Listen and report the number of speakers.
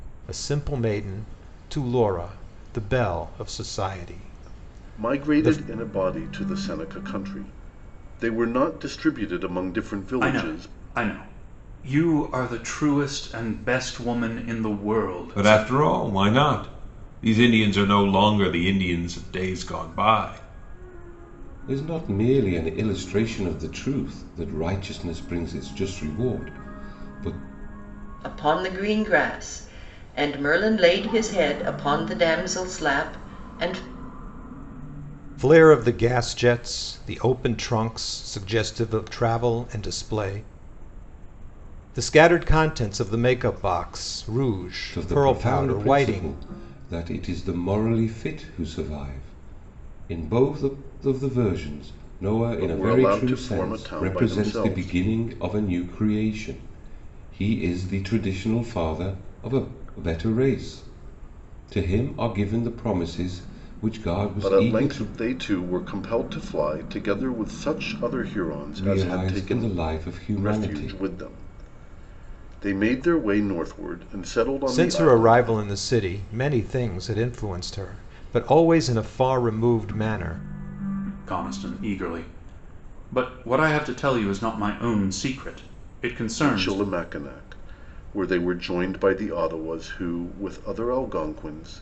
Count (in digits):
6